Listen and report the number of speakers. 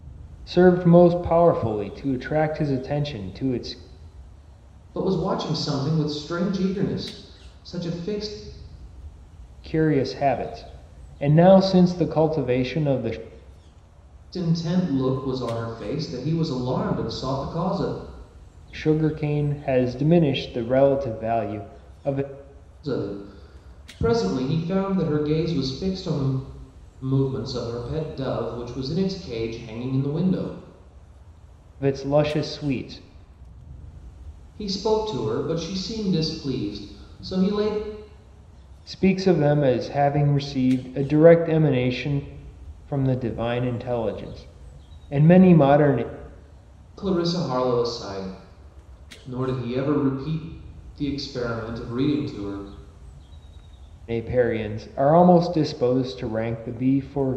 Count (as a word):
two